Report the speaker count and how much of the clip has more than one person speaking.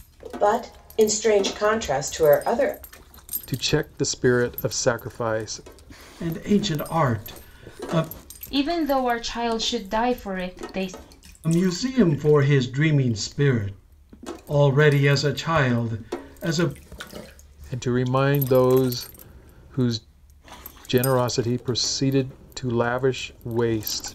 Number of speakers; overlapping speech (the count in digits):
4, no overlap